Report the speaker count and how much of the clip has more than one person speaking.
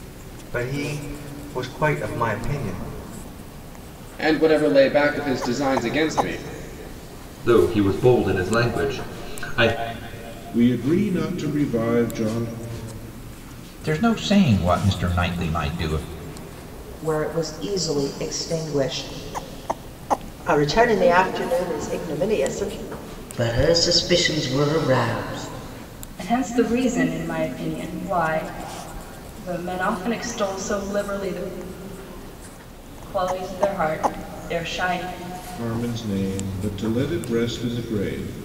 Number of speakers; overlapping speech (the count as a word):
nine, no overlap